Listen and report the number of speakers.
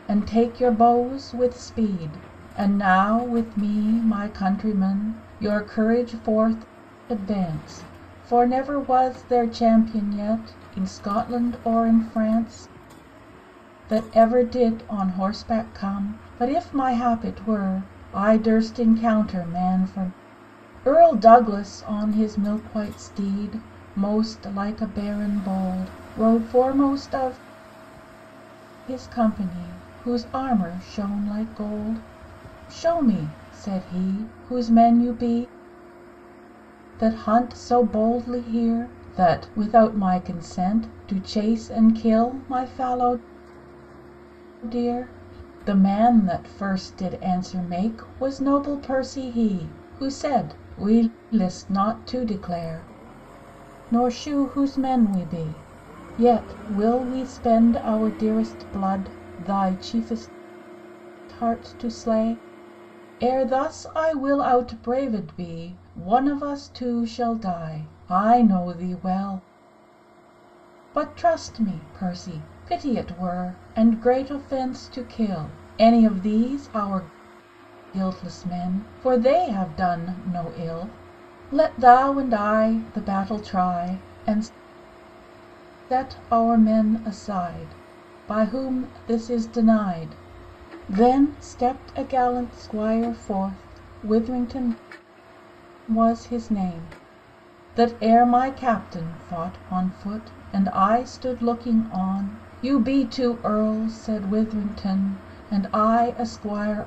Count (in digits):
1